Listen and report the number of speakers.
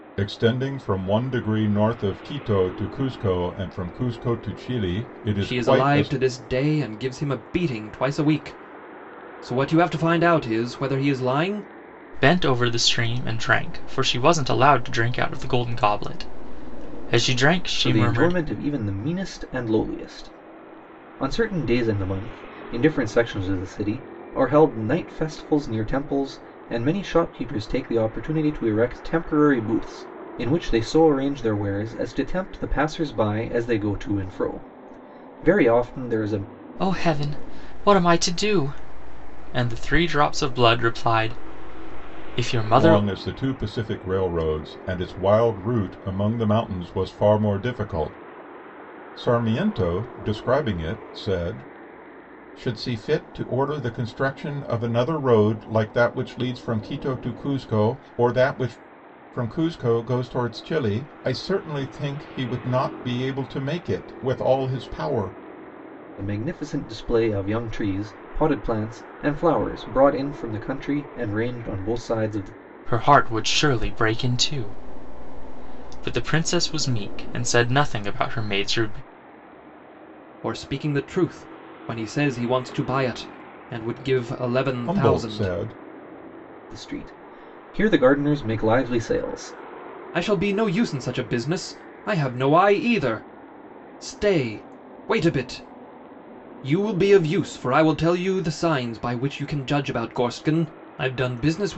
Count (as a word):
four